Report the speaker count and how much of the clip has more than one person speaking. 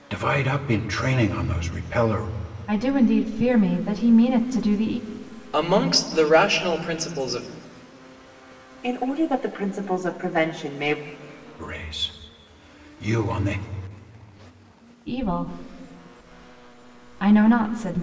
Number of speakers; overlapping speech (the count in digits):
4, no overlap